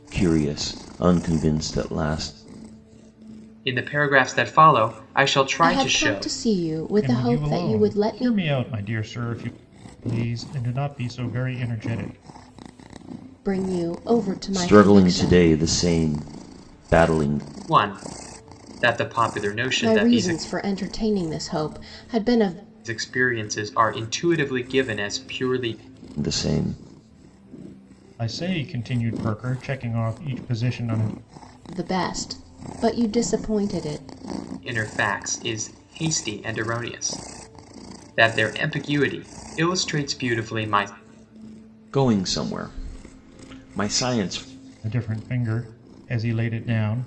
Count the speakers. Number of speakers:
4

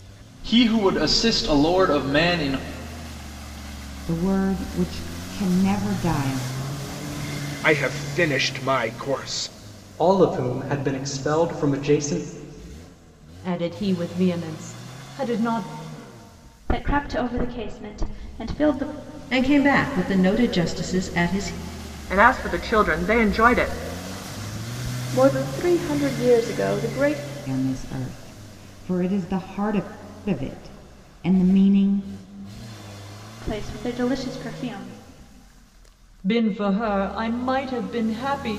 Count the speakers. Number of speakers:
9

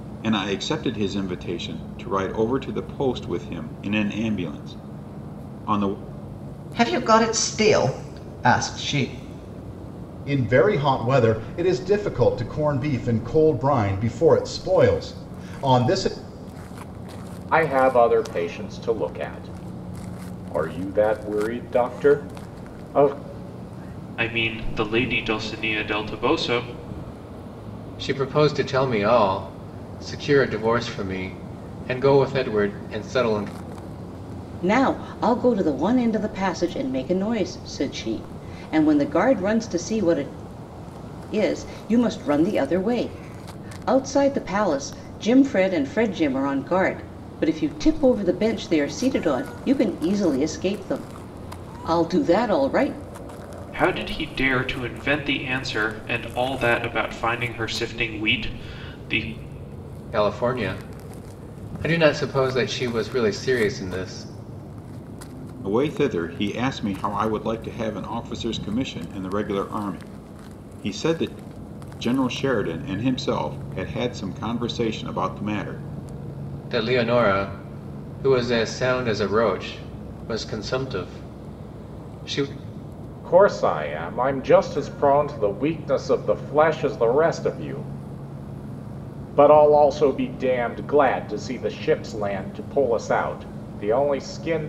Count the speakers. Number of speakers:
7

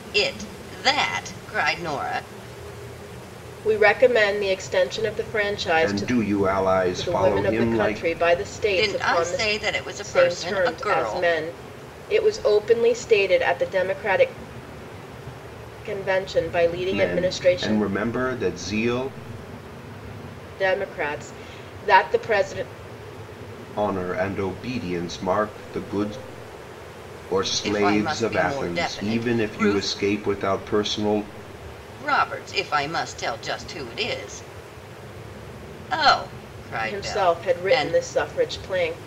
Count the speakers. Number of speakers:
3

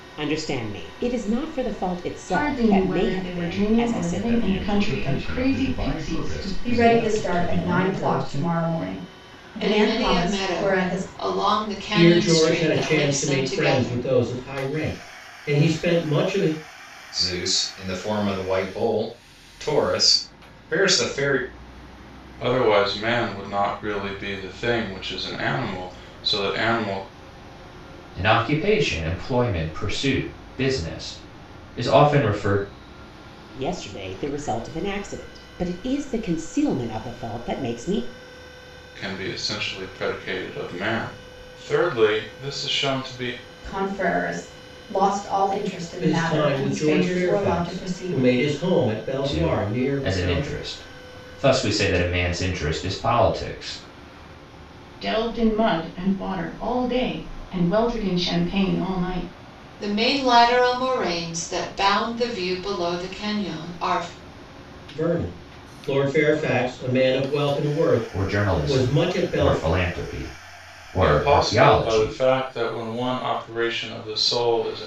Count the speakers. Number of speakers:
9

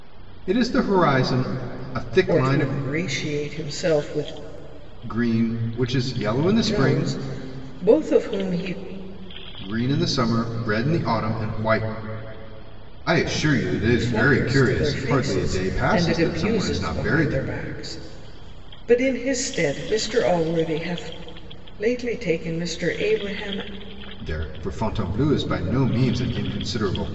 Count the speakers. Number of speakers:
2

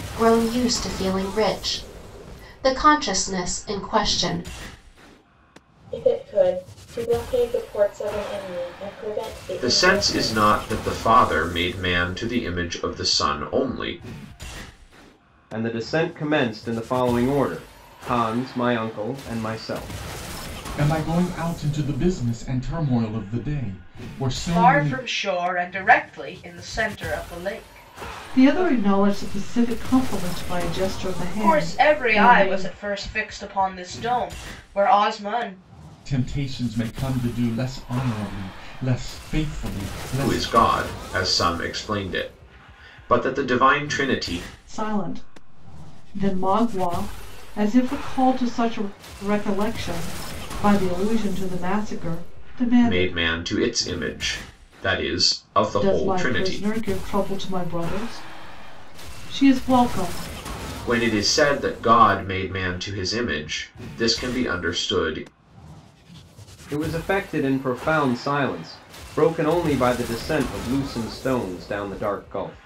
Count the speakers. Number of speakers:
7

